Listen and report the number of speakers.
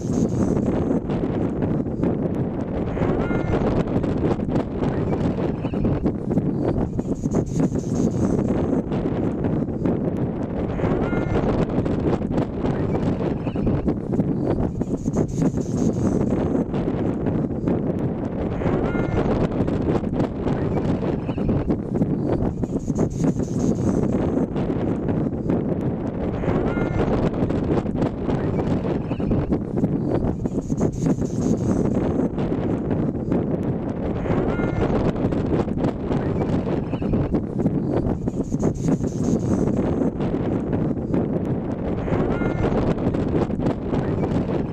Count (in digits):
0